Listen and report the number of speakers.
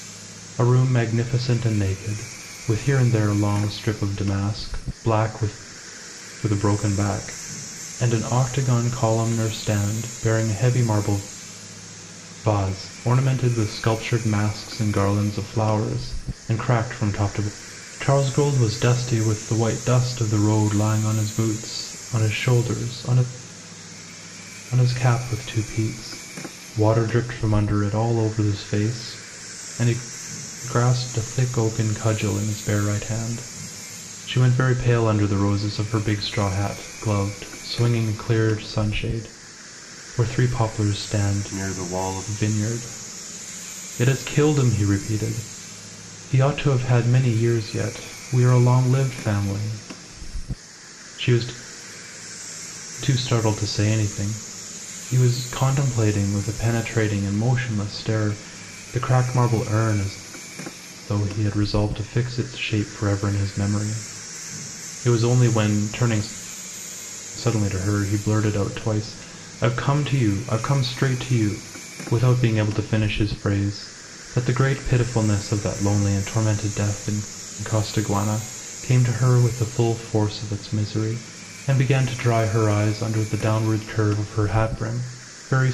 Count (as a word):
one